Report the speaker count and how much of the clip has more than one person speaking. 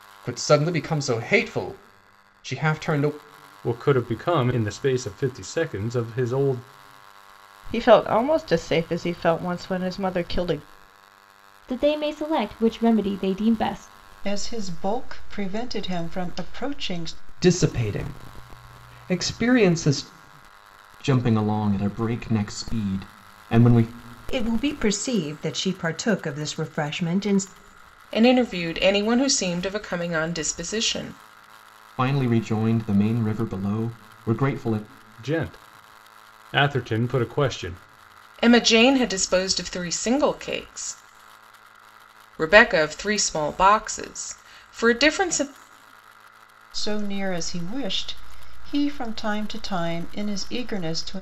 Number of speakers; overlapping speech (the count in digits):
9, no overlap